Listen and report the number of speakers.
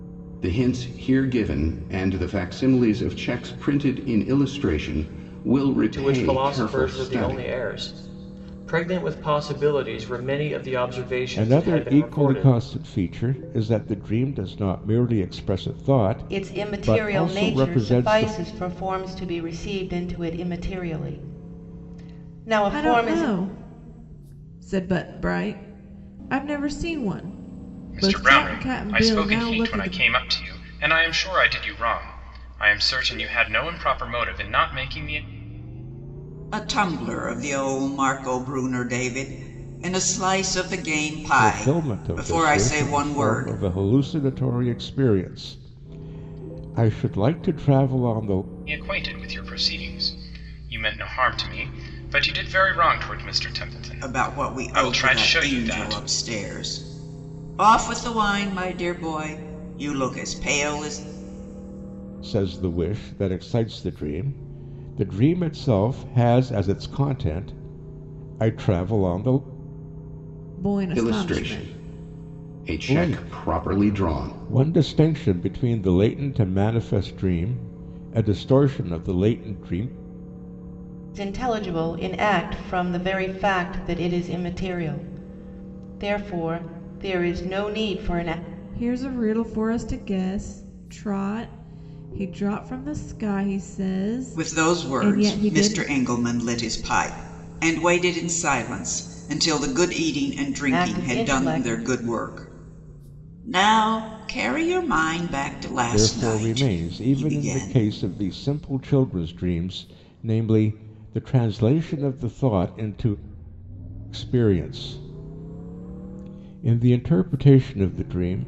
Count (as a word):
seven